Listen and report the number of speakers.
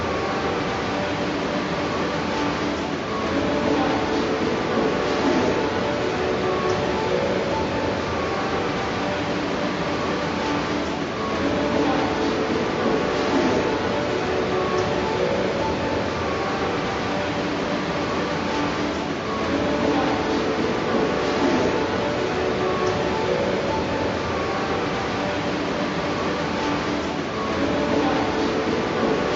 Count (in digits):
0